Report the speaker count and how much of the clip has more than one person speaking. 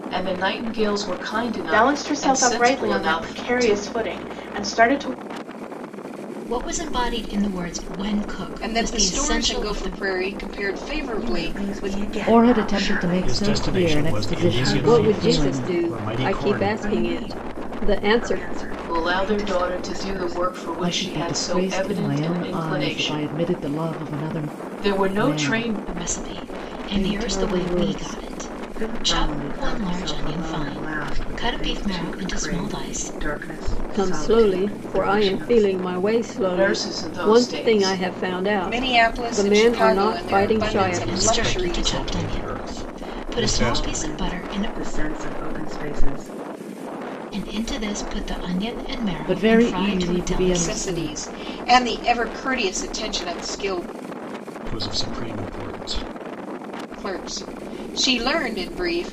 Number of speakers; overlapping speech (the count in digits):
8, about 58%